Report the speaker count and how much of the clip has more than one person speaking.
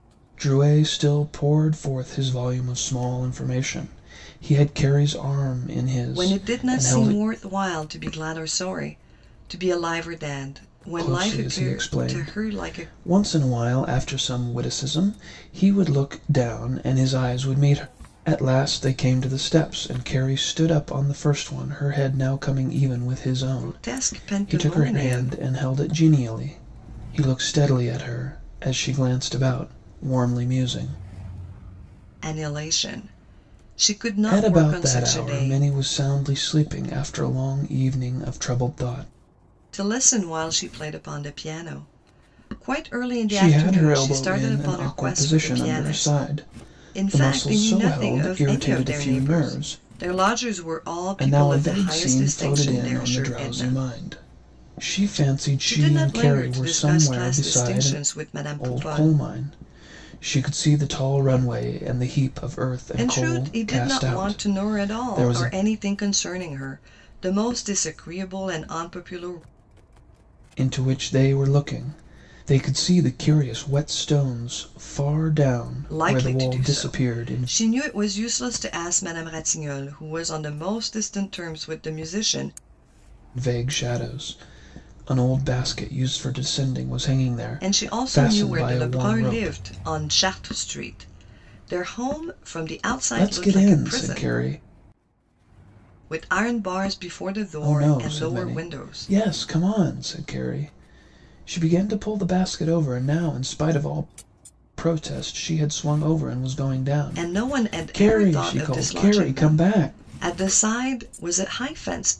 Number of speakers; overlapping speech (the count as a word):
two, about 27%